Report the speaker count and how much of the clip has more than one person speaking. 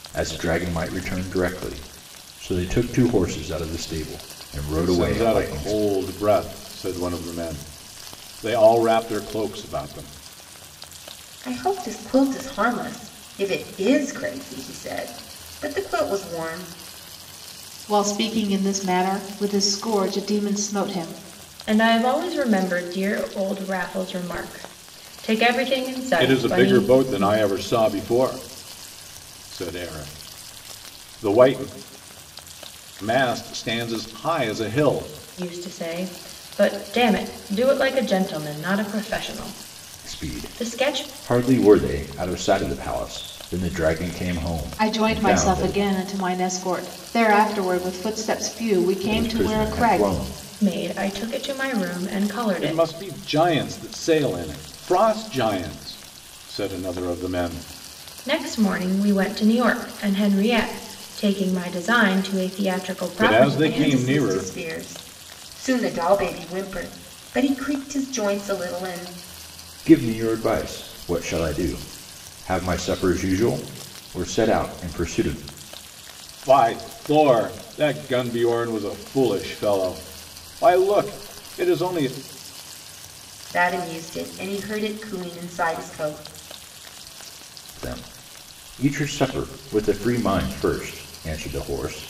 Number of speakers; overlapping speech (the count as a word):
five, about 8%